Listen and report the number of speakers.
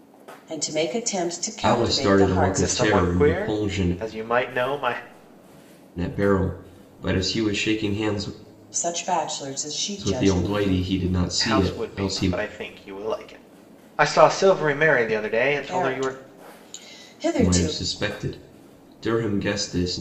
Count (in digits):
3